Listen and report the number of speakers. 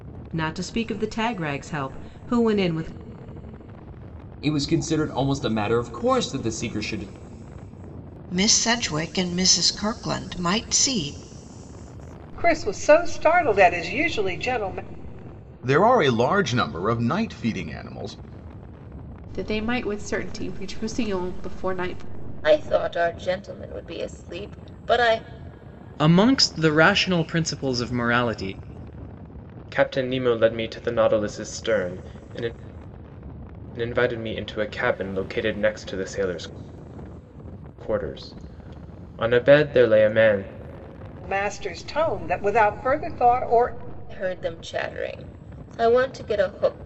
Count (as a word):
nine